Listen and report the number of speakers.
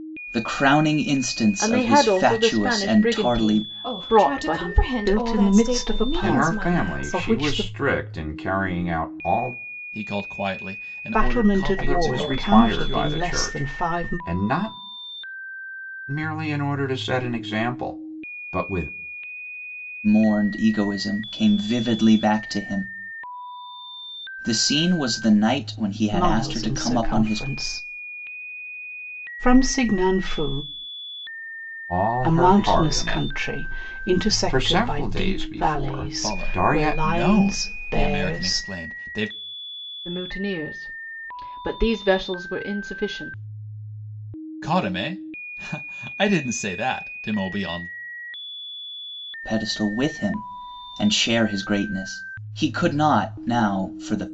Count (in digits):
6